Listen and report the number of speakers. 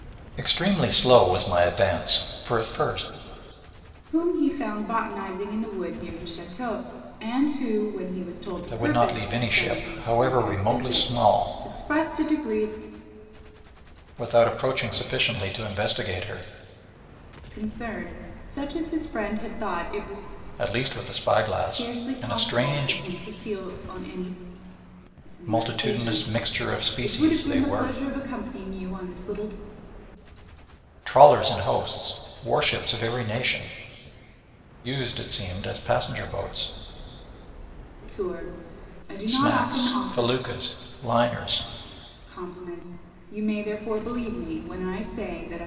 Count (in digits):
2